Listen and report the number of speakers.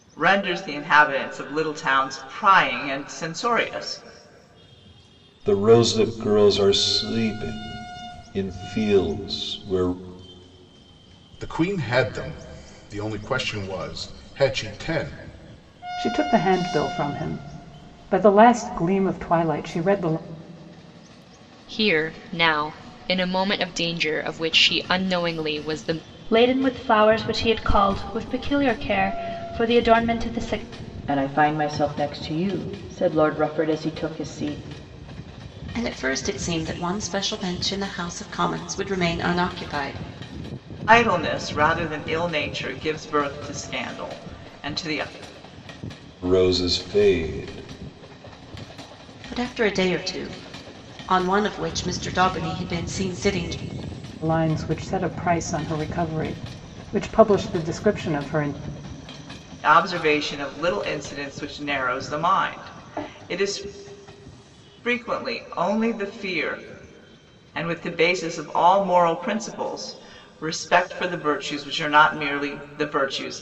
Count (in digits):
8